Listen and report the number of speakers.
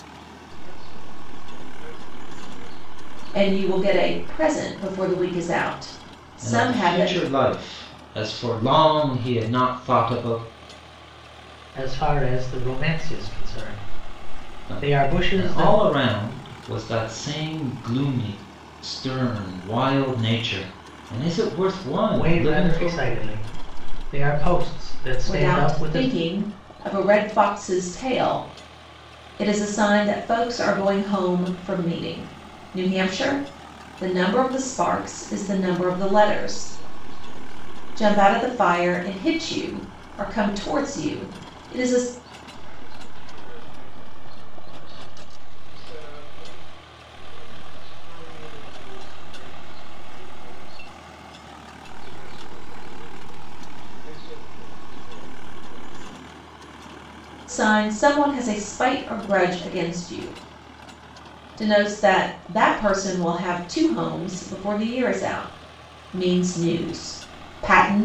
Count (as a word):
four